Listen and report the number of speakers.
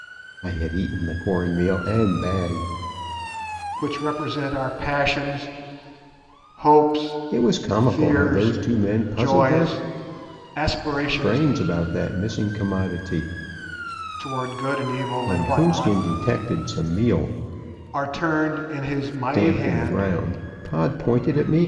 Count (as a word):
two